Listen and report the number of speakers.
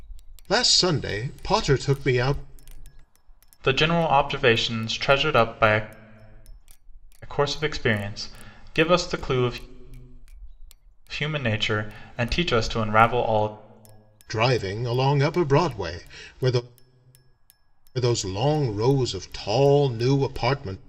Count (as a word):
two